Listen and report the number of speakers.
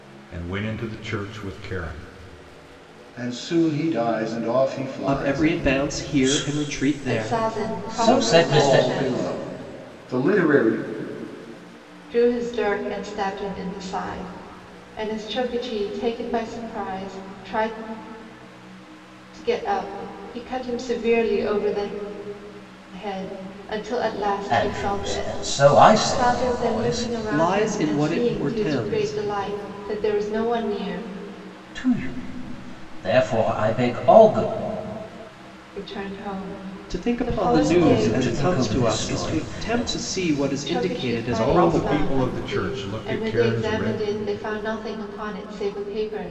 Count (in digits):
5